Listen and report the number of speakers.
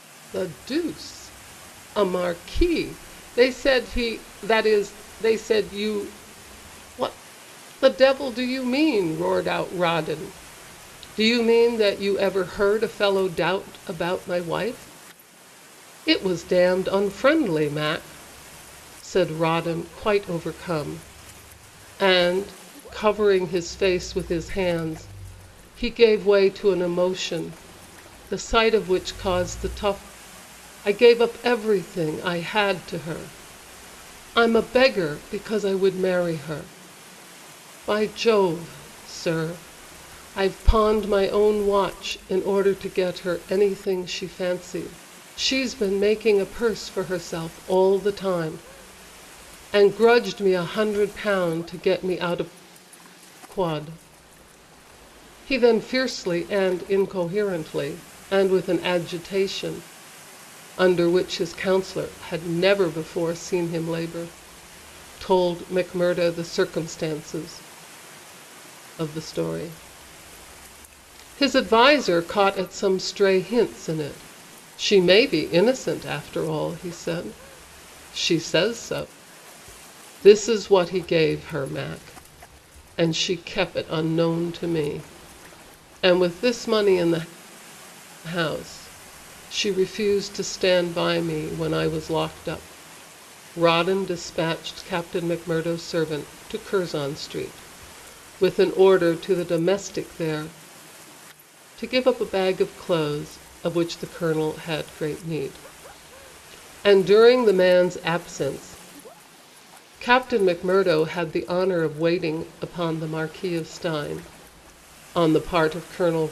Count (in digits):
1